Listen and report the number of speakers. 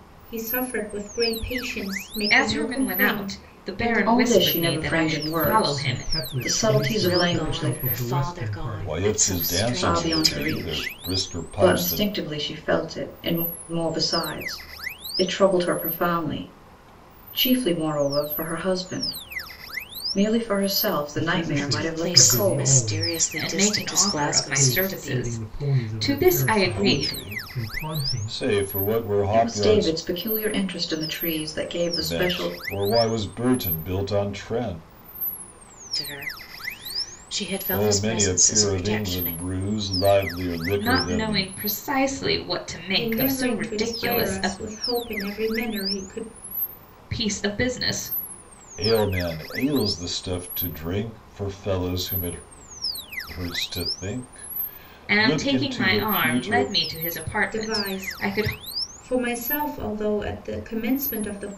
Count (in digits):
6